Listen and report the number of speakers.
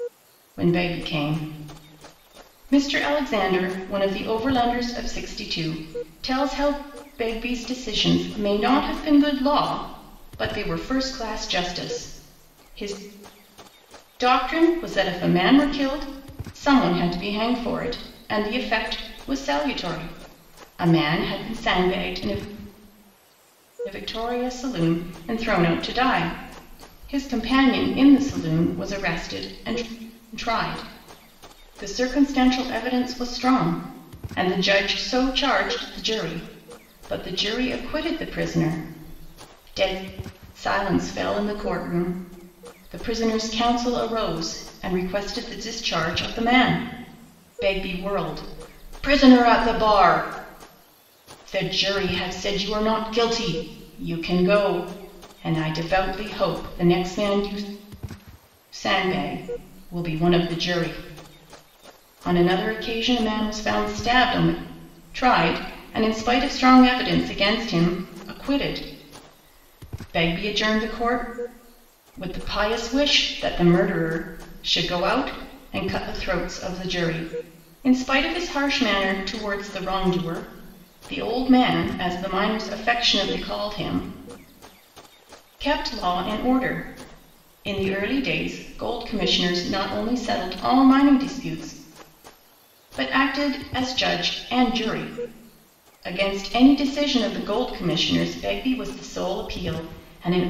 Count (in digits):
1